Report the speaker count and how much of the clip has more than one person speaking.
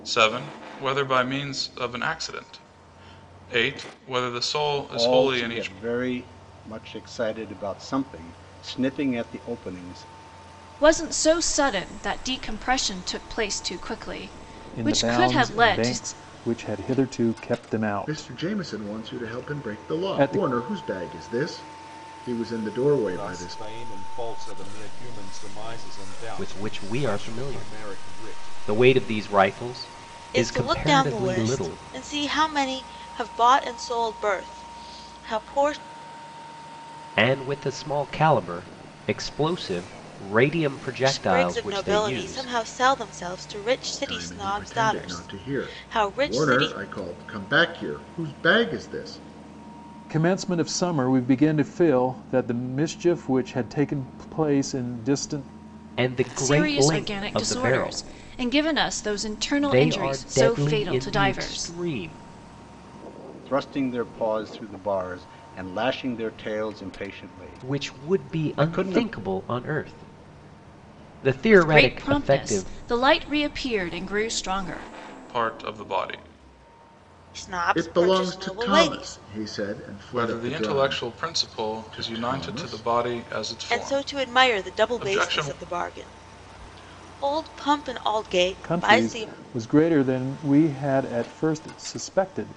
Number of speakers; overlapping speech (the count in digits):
8, about 29%